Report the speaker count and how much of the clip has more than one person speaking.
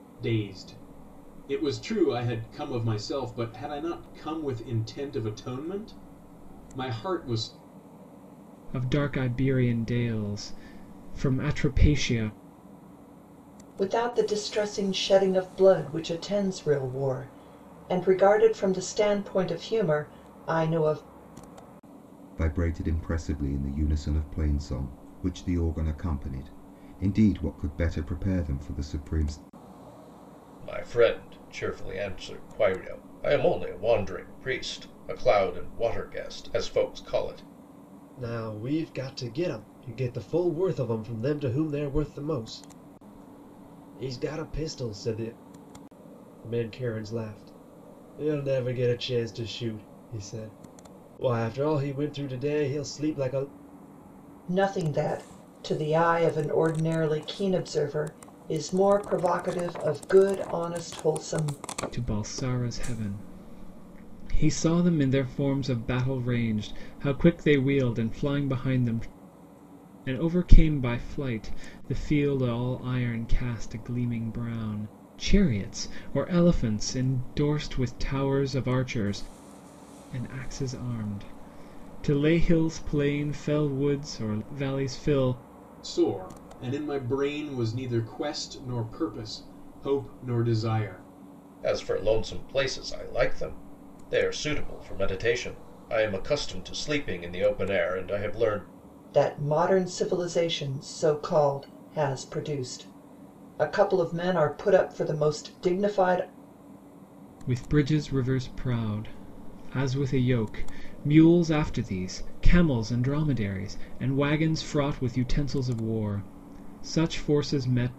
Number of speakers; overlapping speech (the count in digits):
6, no overlap